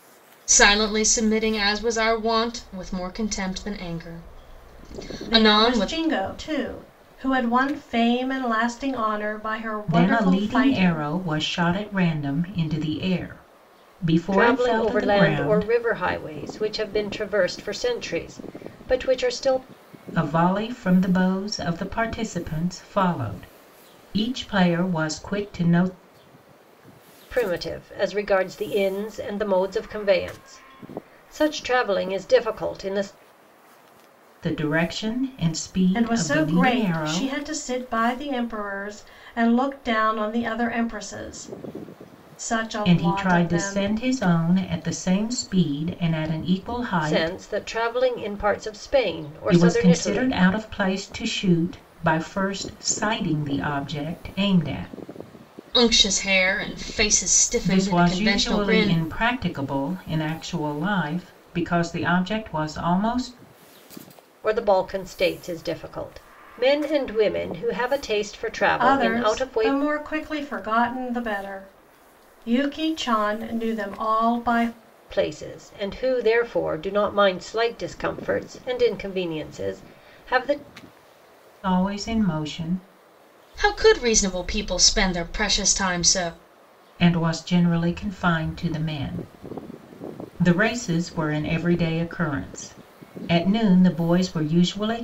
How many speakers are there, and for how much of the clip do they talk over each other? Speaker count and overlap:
four, about 10%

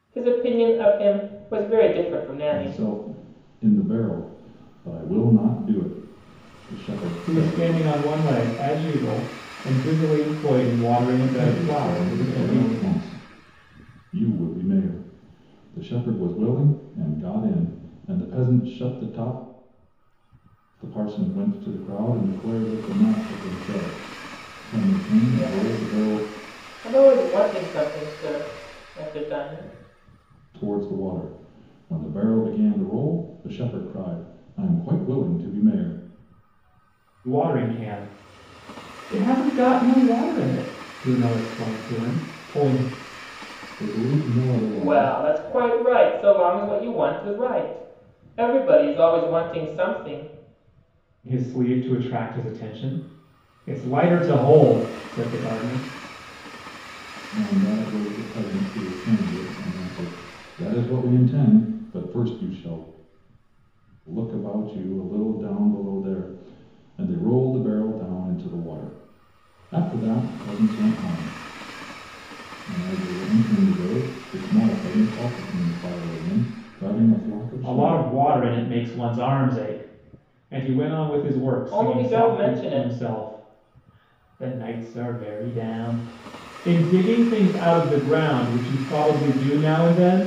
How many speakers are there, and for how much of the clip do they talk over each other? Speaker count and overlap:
three, about 6%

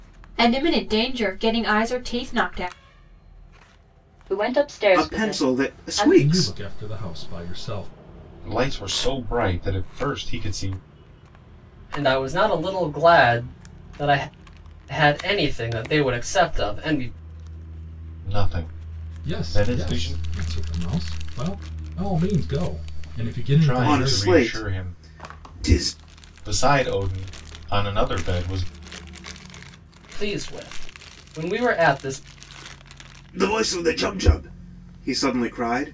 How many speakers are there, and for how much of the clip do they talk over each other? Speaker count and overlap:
six, about 11%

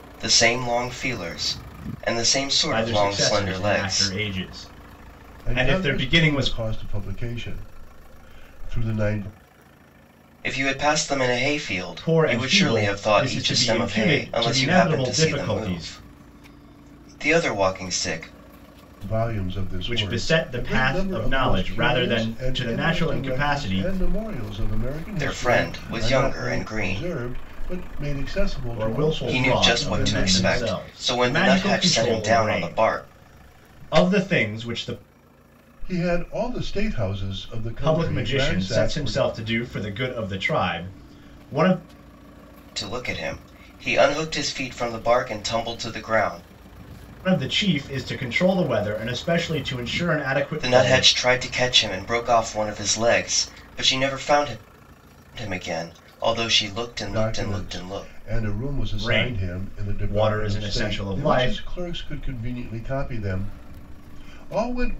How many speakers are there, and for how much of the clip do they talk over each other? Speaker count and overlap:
three, about 35%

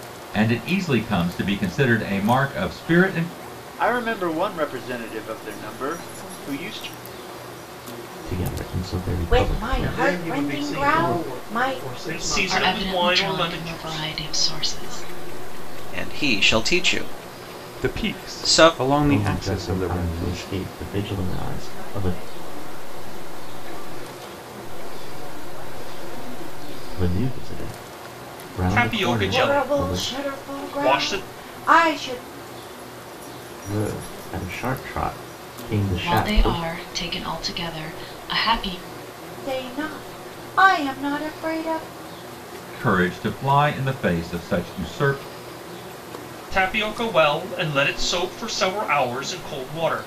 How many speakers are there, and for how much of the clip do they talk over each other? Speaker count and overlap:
ten, about 28%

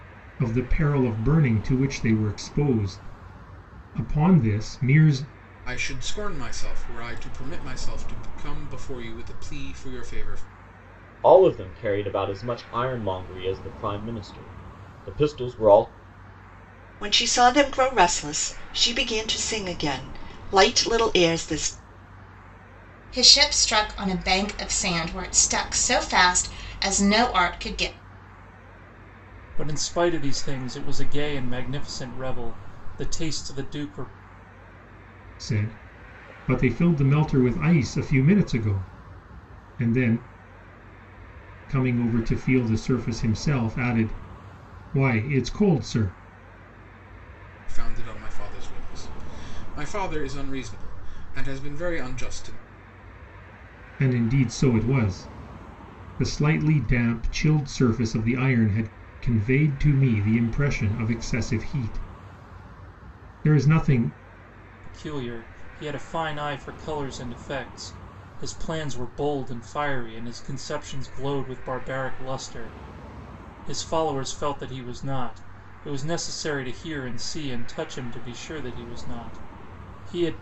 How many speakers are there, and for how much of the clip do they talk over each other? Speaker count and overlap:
six, no overlap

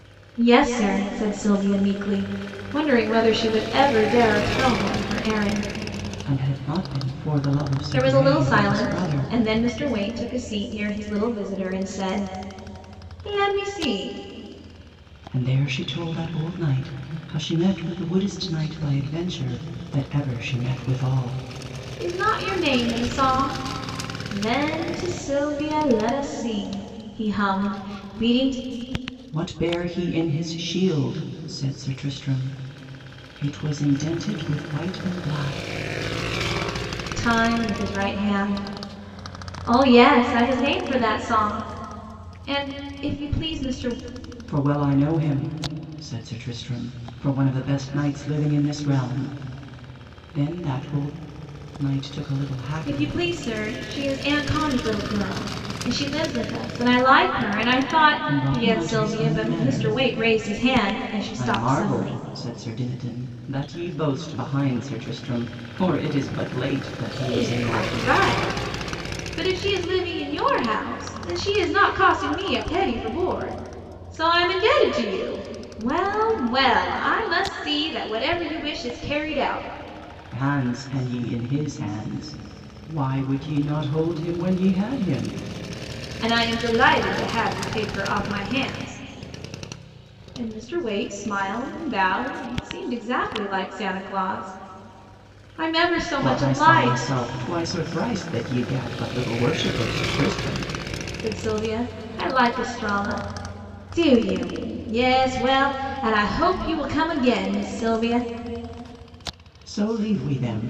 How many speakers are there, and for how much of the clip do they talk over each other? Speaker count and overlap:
two, about 6%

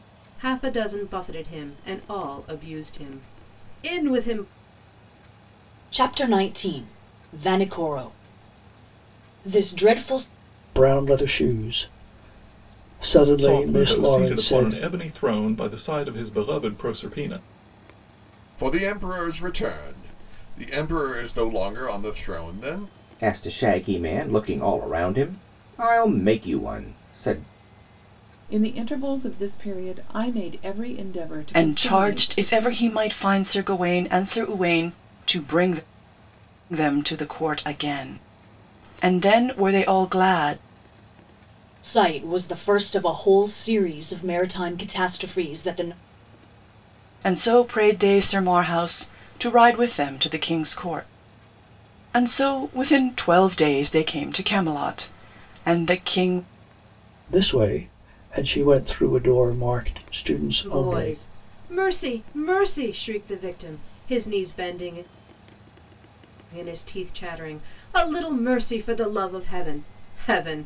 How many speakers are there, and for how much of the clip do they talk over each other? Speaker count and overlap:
eight, about 5%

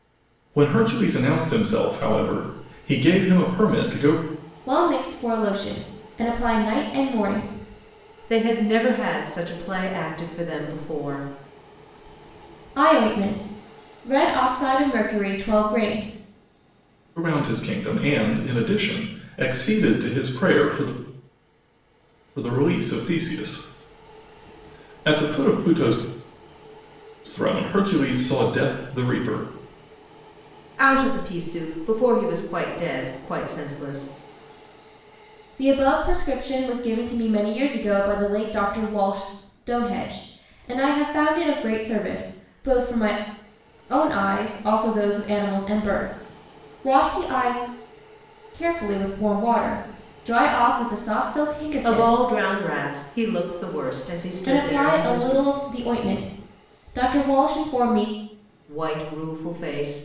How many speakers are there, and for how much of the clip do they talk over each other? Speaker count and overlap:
three, about 2%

